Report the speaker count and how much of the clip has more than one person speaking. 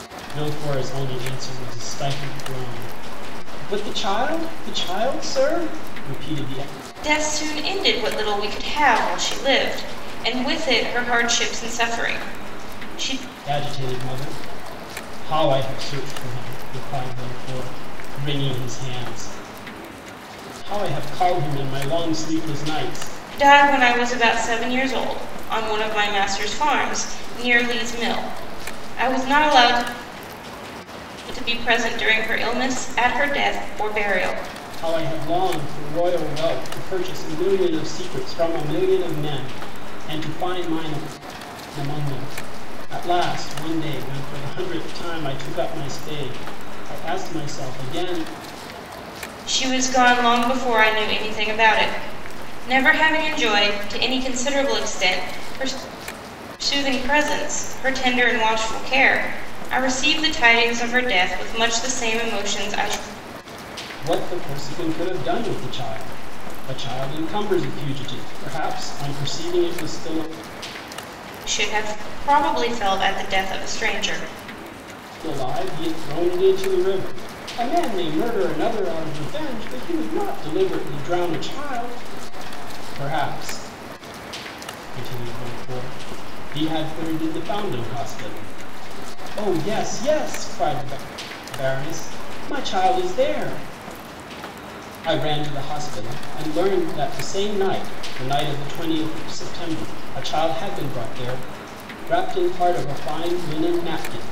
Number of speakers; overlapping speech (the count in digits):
2, no overlap